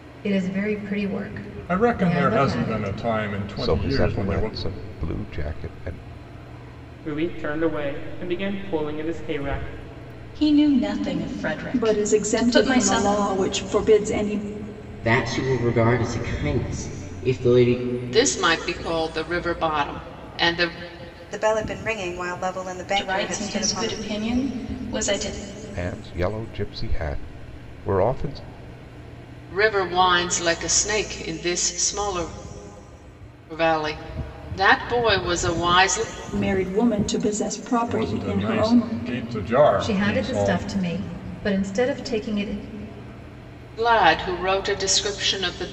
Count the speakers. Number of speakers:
9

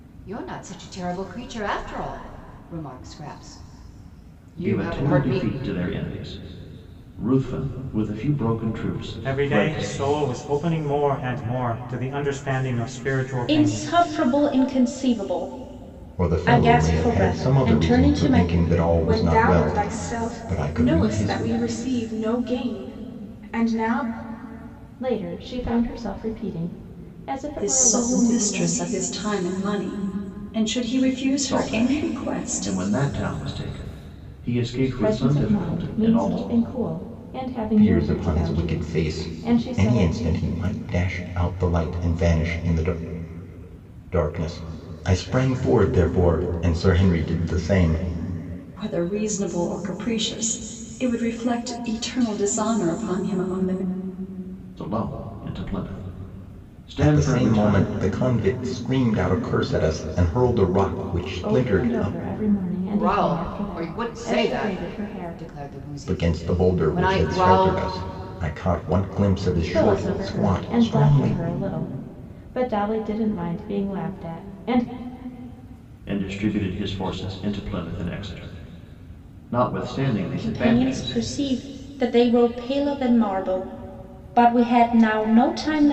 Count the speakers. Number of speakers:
8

